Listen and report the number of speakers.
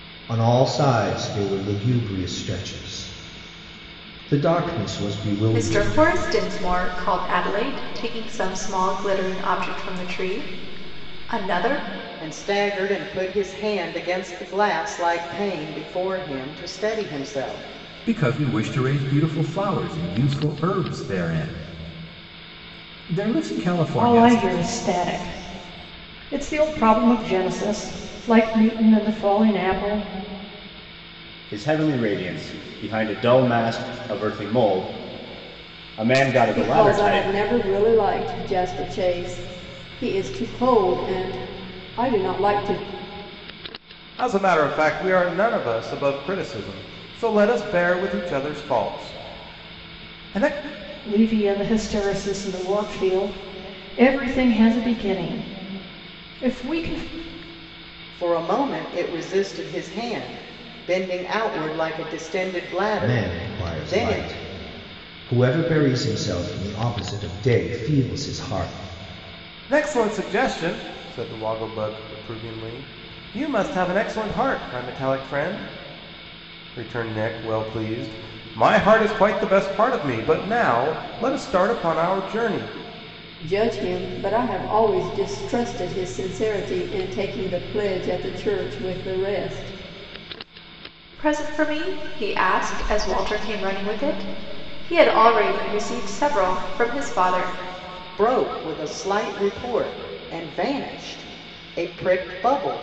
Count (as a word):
eight